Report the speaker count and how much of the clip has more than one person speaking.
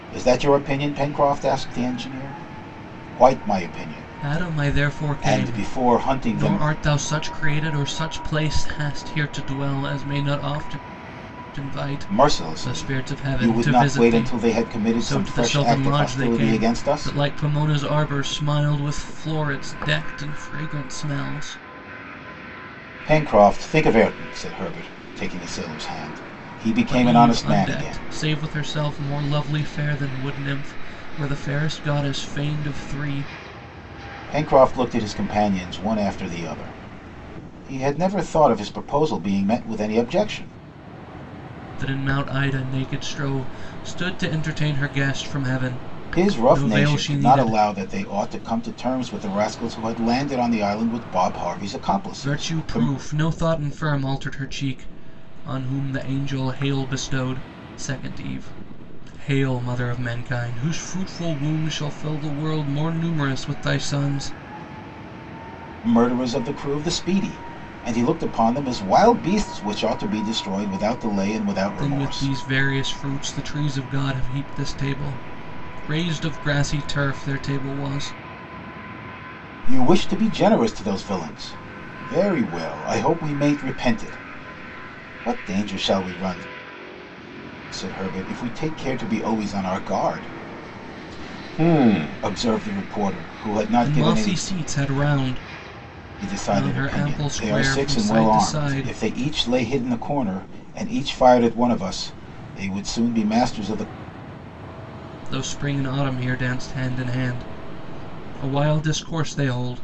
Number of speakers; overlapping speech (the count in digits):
2, about 13%